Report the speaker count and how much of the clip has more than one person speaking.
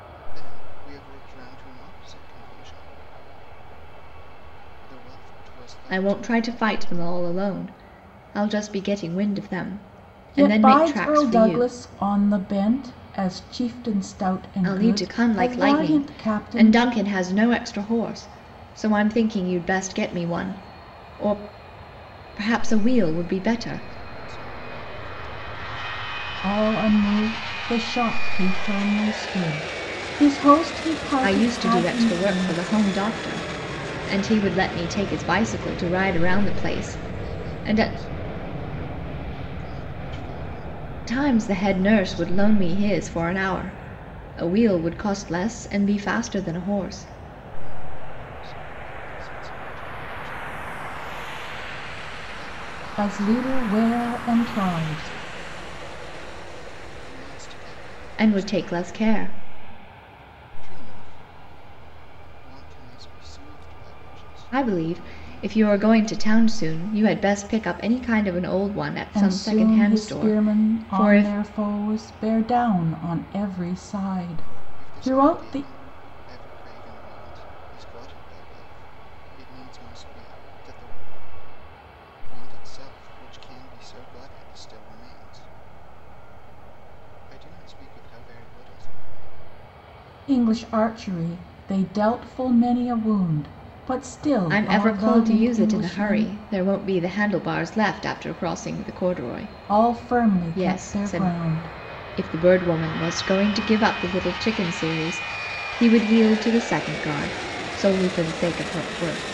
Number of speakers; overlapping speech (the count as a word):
three, about 22%